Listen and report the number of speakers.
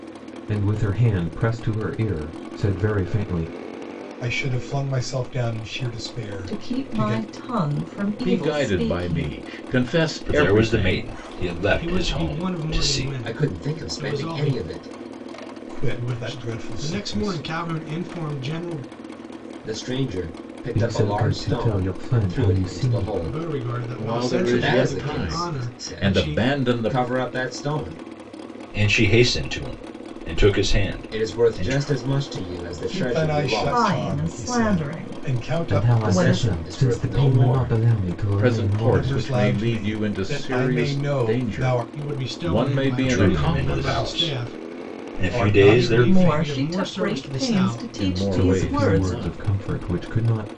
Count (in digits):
7